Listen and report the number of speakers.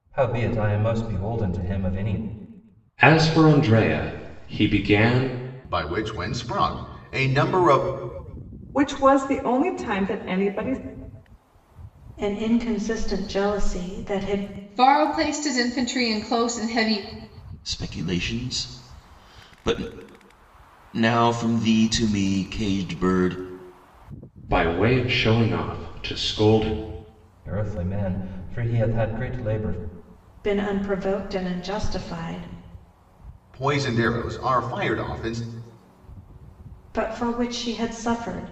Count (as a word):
seven